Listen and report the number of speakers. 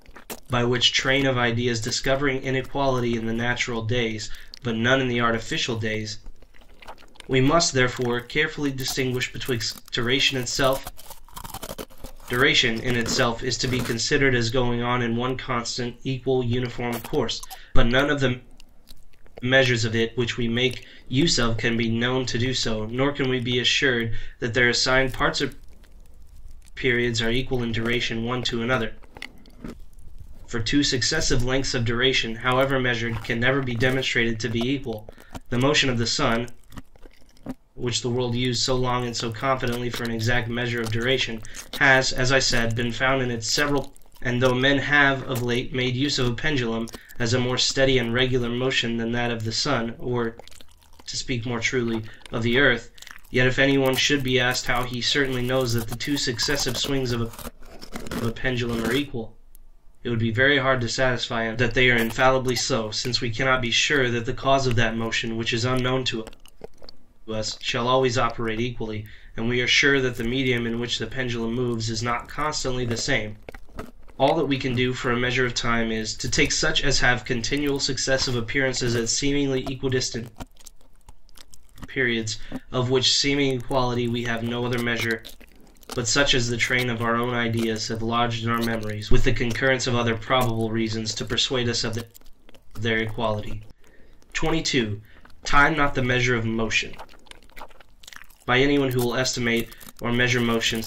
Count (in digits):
1